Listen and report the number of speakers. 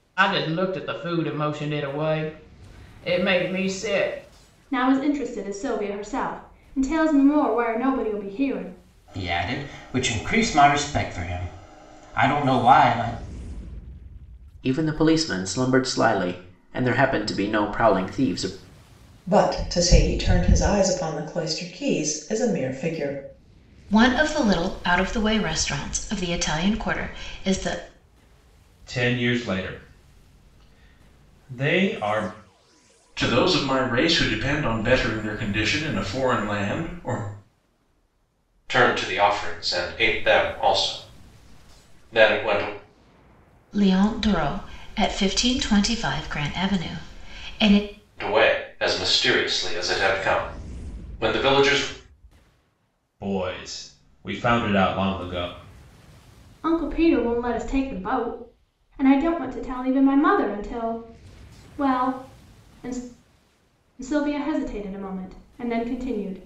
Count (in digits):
9